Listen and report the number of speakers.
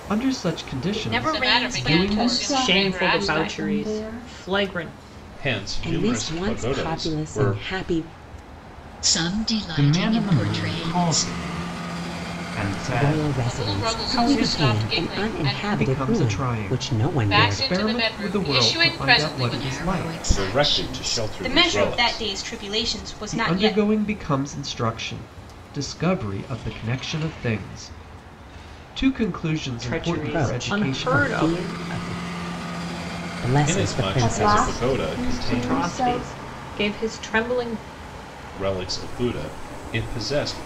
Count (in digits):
9